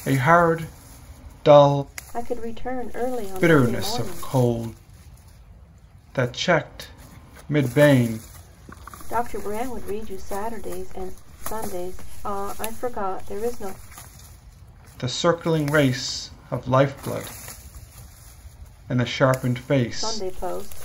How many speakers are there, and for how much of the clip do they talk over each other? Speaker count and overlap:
two, about 6%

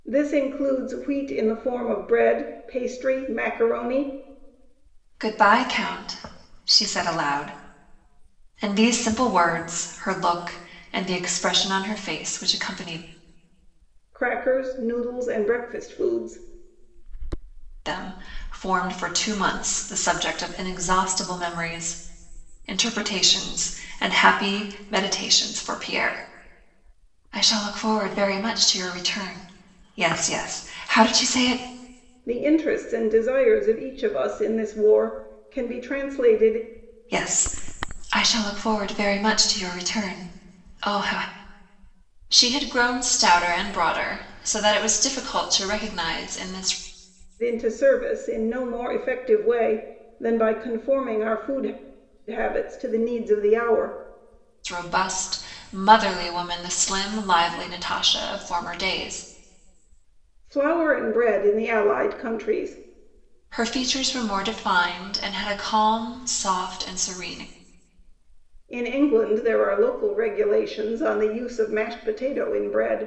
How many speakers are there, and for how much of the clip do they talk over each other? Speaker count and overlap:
two, no overlap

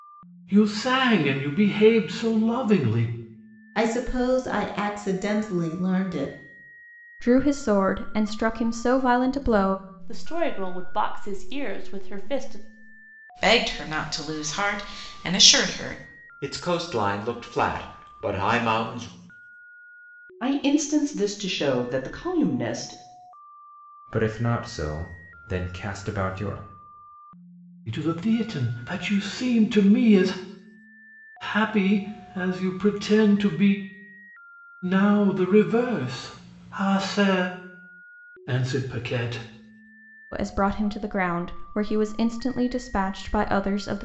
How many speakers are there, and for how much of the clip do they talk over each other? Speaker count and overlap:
eight, no overlap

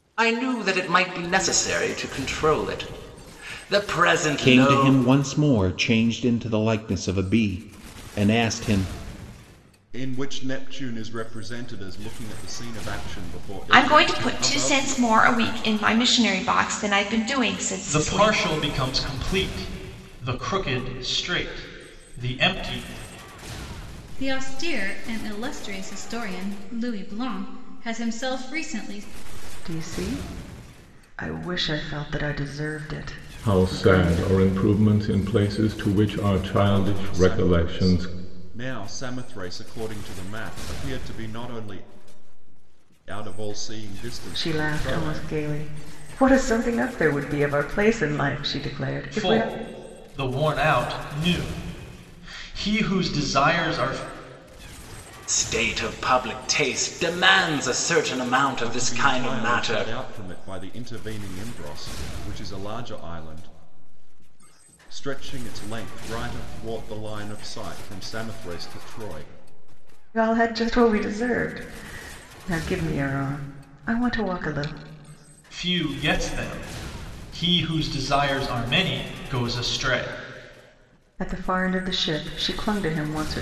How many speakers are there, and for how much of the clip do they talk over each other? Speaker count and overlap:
eight, about 9%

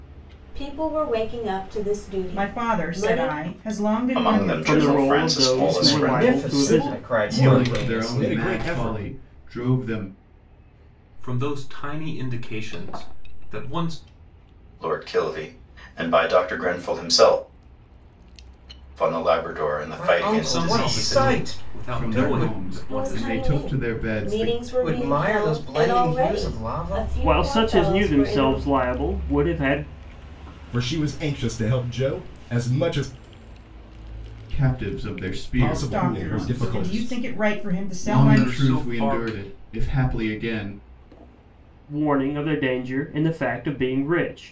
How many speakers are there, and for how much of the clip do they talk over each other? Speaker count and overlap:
eight, about 41%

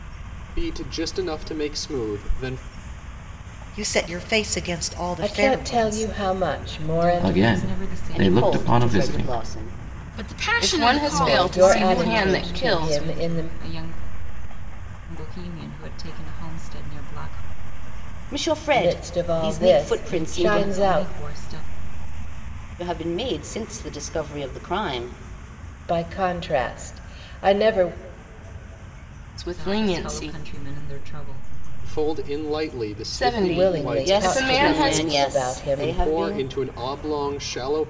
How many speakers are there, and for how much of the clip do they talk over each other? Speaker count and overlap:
eight, about 34%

